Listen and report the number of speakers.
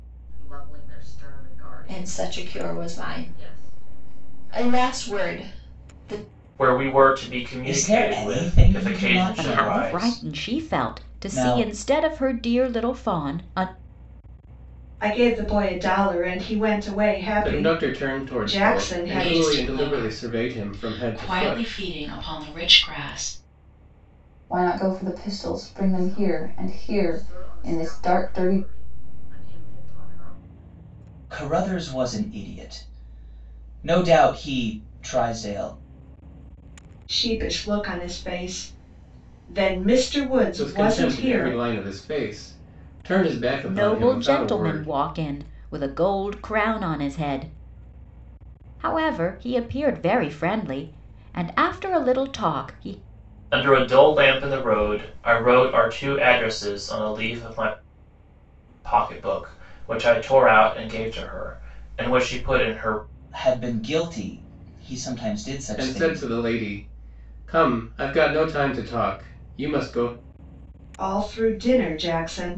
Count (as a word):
nine